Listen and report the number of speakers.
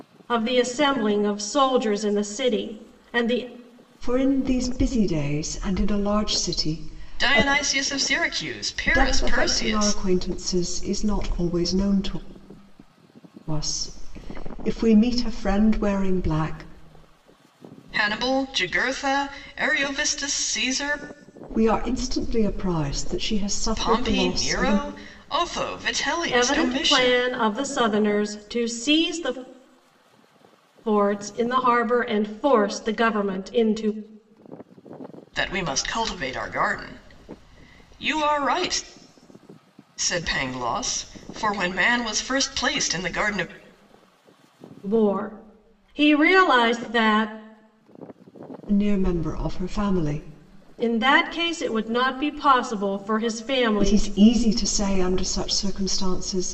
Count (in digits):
3